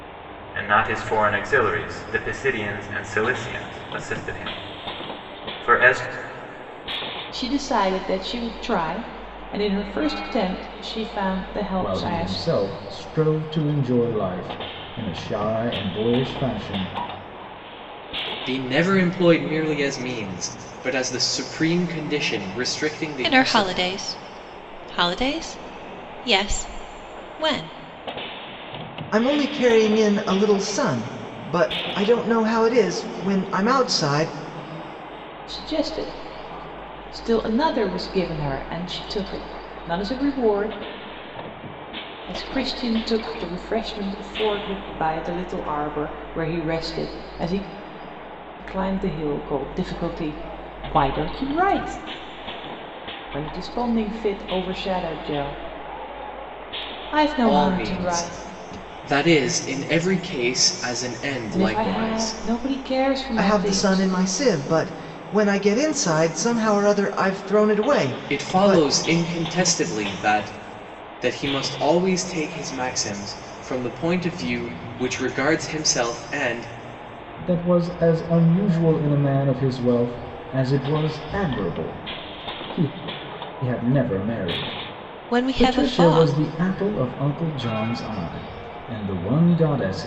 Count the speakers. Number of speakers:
6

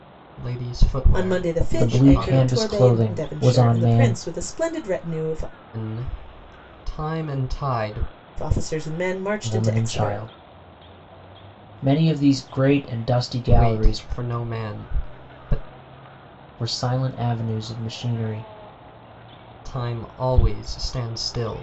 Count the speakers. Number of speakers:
3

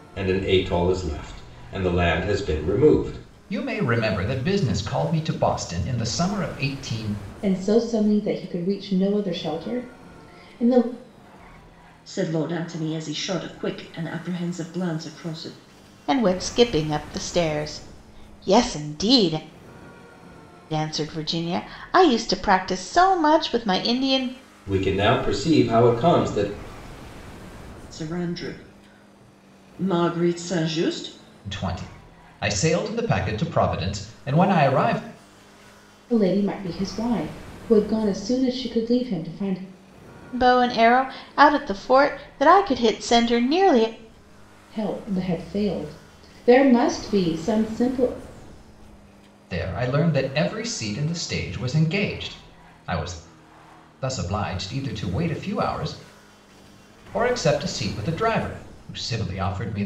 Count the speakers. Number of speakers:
5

